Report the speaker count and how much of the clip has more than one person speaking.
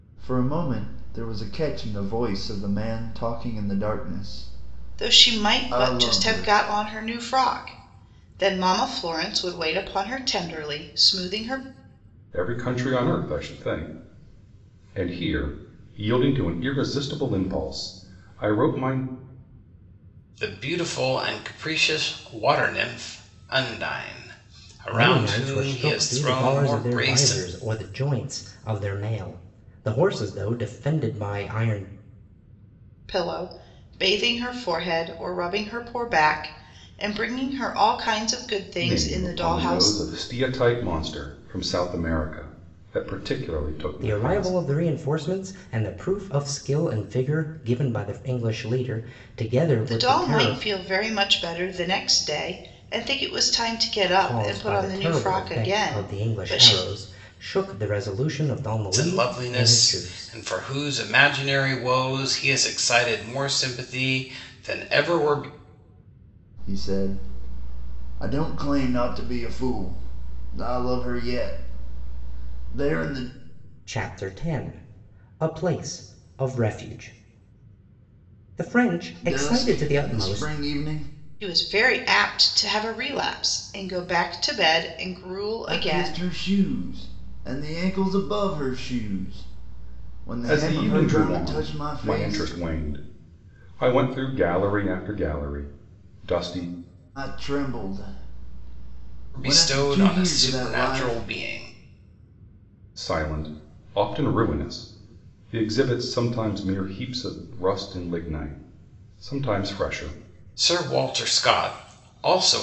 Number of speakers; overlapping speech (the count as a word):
five, about 15%